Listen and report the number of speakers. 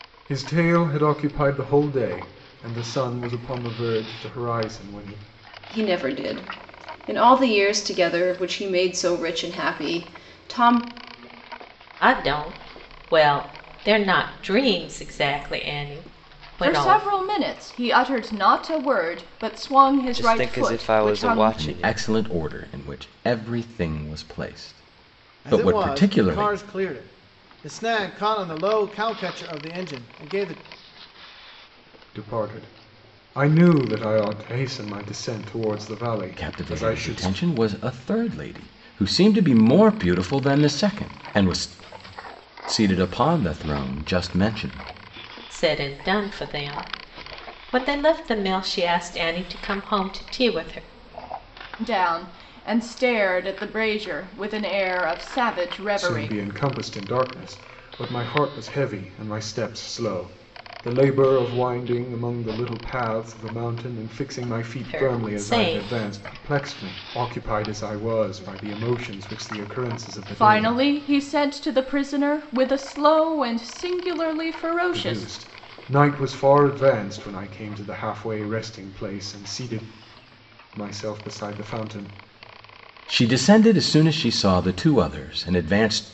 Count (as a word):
seven